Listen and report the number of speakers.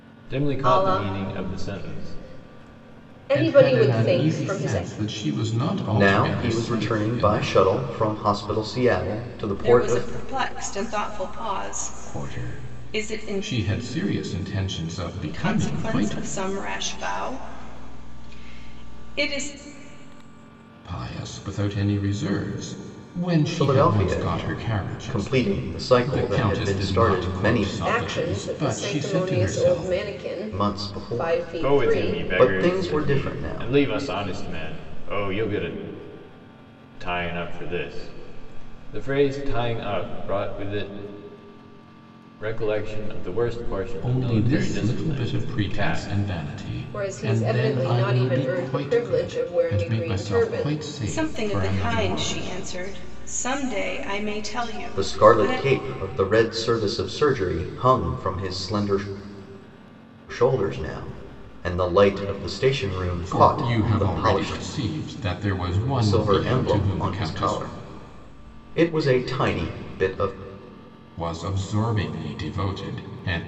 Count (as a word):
five